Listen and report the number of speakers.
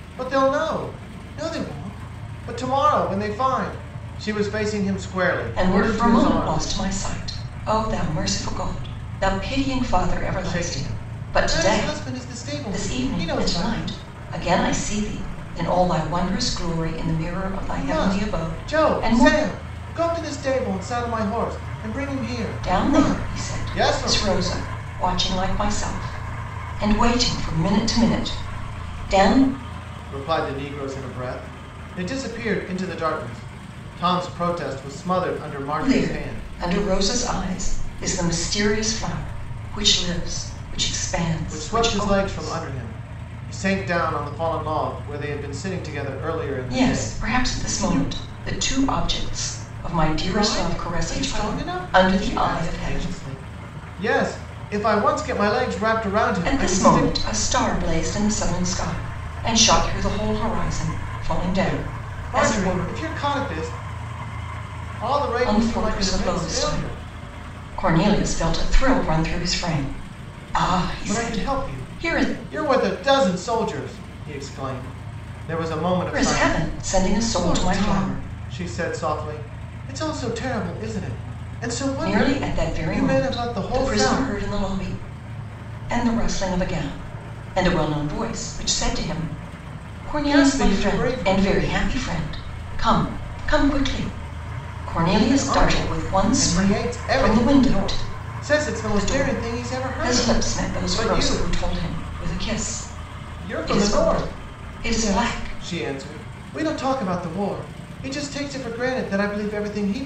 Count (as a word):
two